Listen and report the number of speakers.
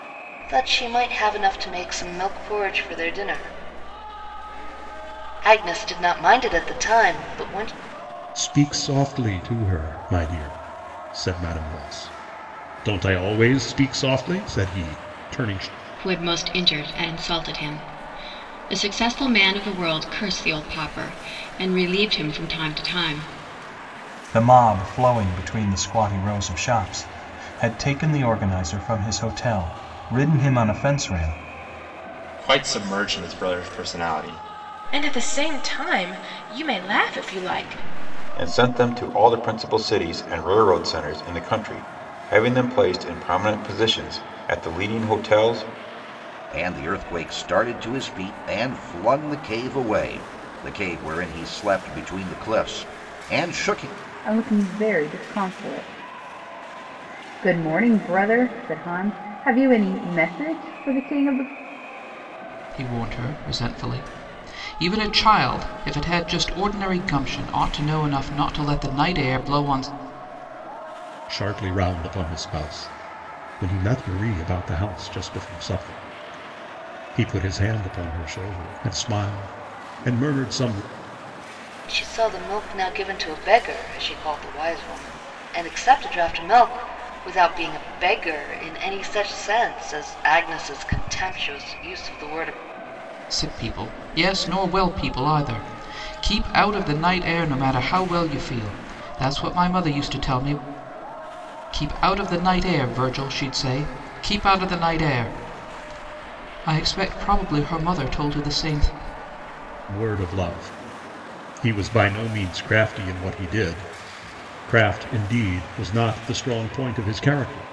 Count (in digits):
10